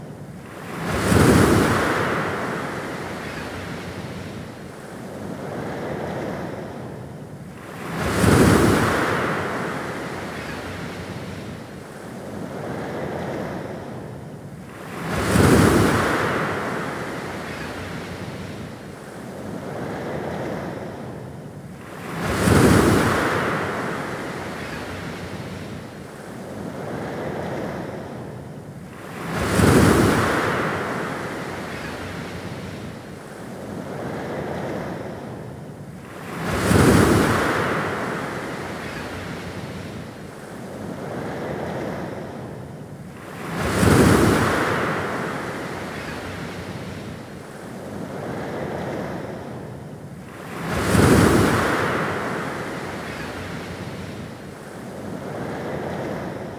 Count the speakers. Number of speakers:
zero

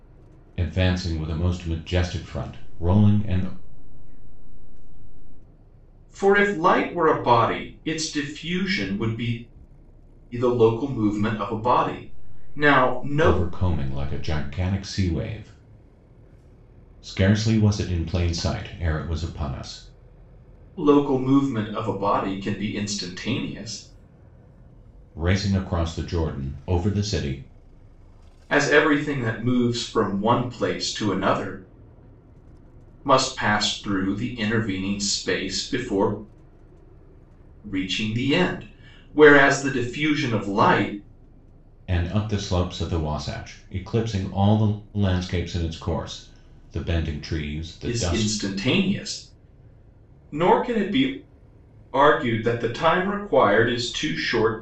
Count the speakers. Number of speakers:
three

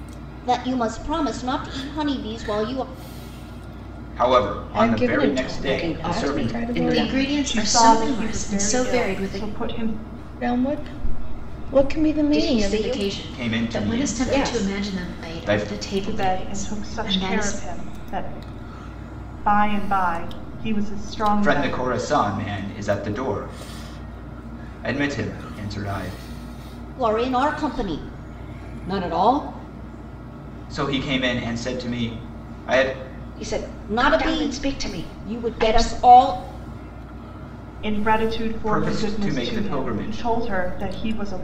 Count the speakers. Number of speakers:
six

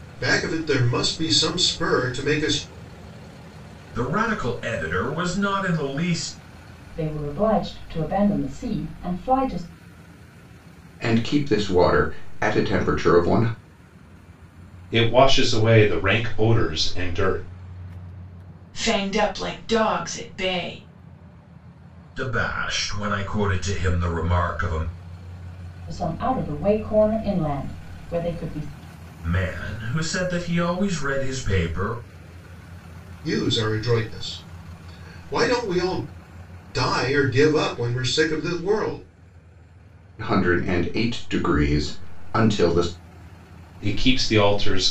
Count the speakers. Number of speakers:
six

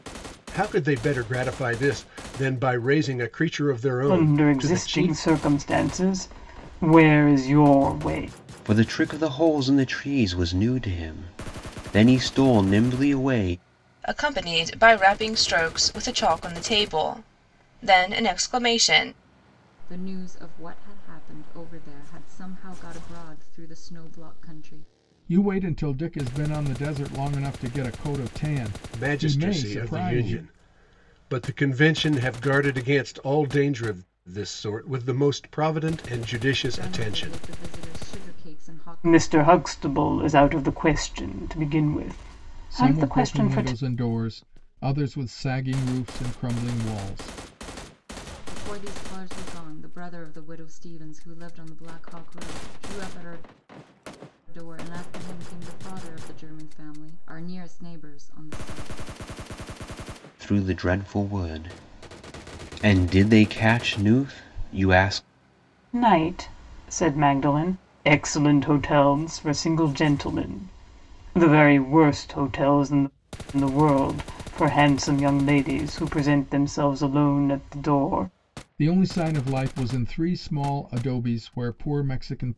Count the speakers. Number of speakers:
six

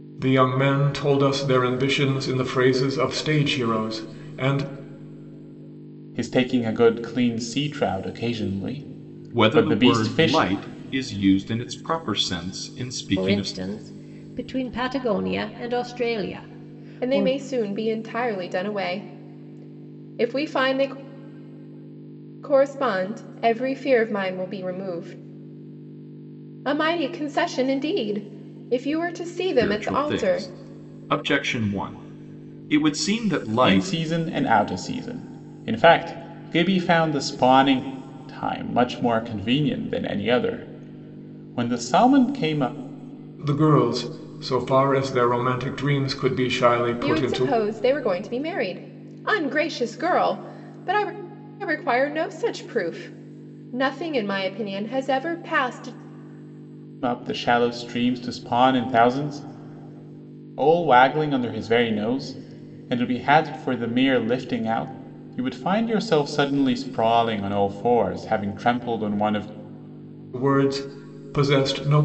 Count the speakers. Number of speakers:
five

